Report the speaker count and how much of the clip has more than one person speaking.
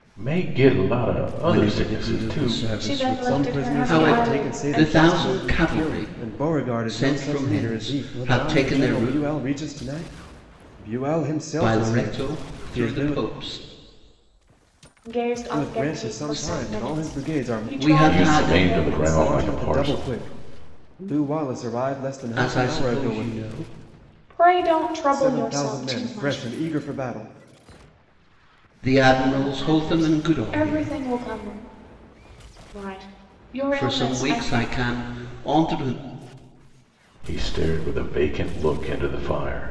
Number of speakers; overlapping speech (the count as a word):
four, about 46%